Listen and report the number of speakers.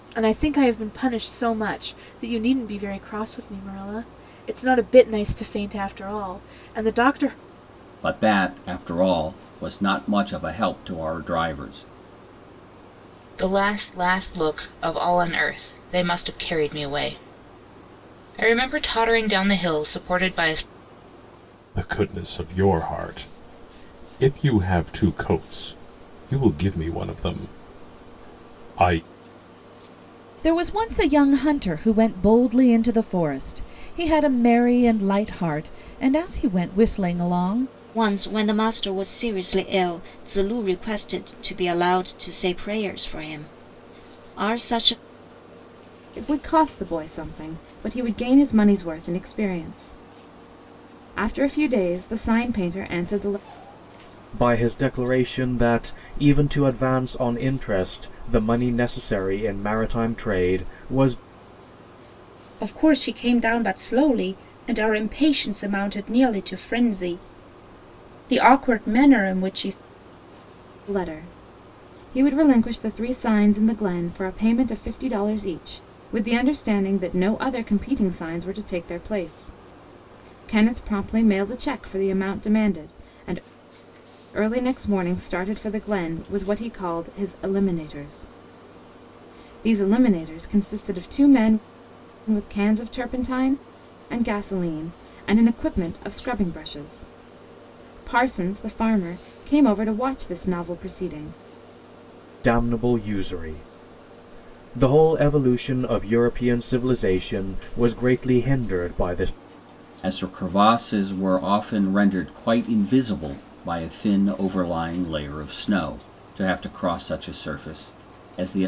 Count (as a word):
nine